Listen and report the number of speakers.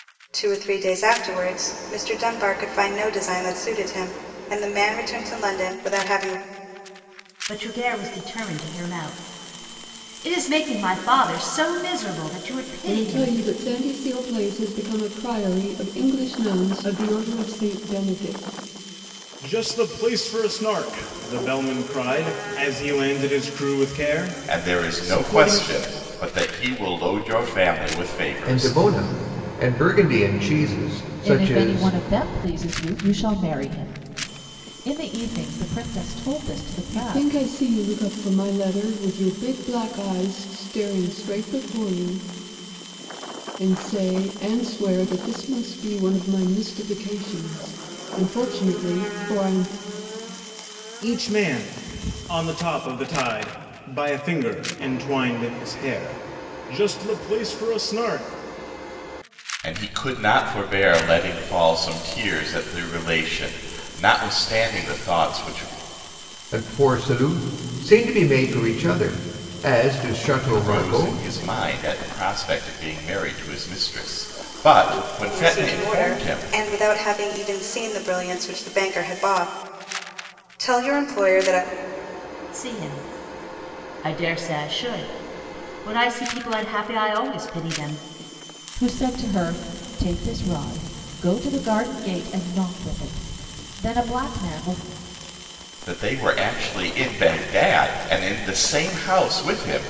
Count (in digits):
7